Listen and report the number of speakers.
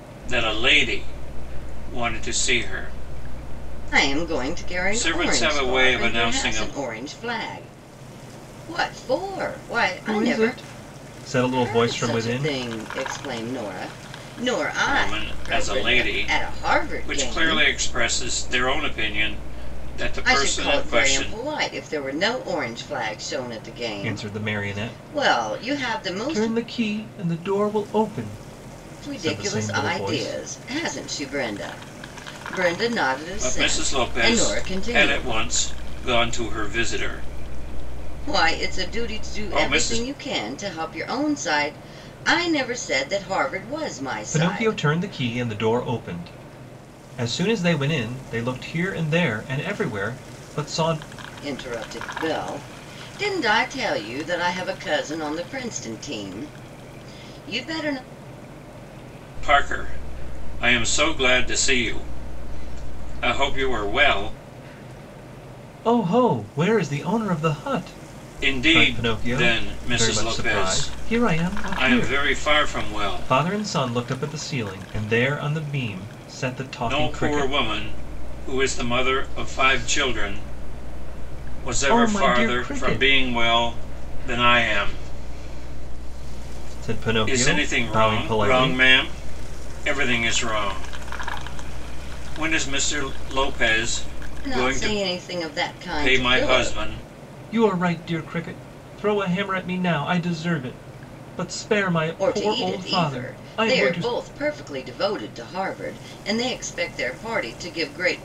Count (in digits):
3